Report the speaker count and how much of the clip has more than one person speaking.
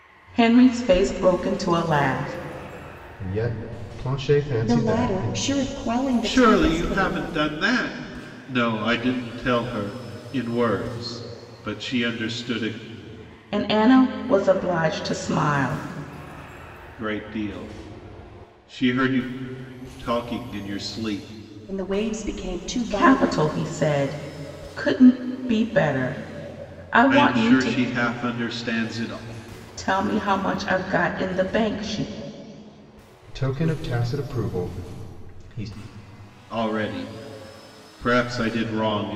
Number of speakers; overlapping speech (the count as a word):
four, about 8%